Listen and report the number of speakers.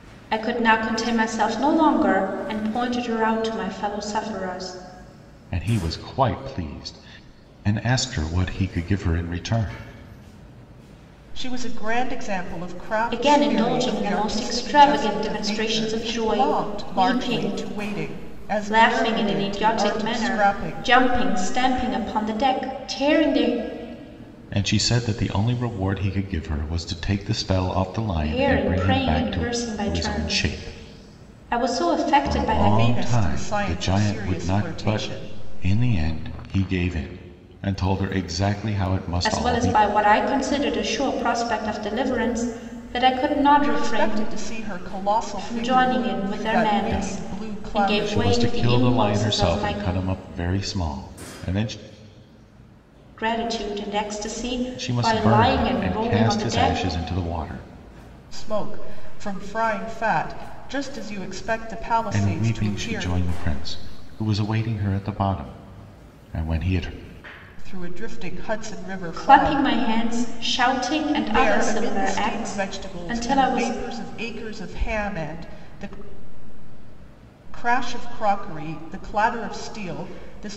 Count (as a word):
three